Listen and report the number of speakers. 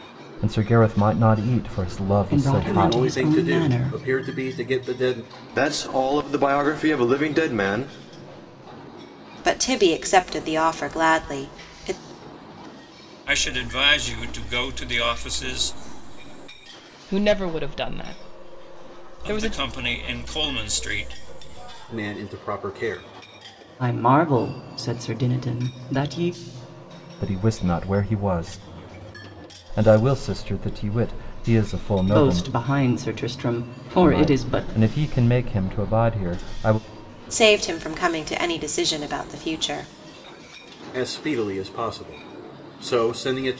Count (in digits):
7